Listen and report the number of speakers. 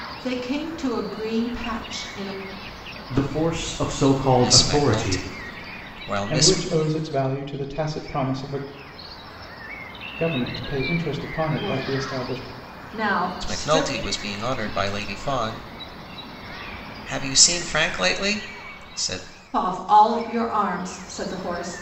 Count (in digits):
4